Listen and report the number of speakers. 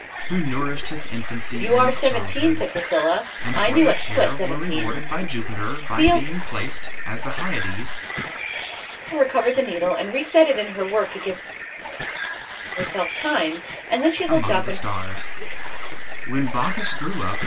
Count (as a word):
two